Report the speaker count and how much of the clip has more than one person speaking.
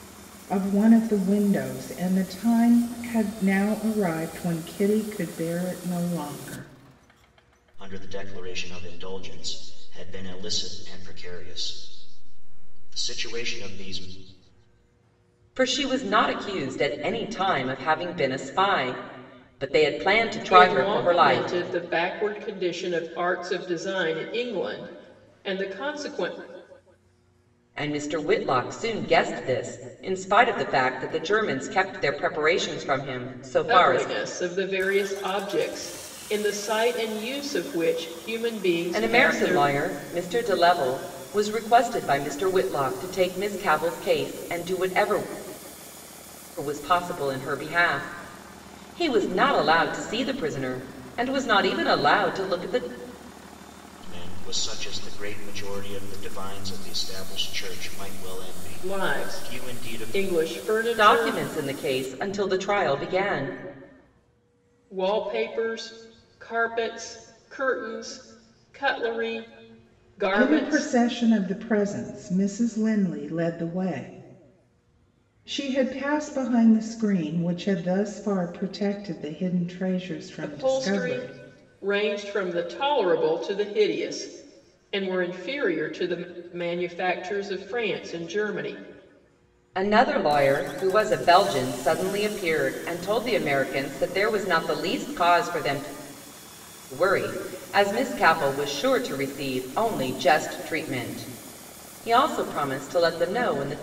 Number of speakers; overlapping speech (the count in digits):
4, about 6%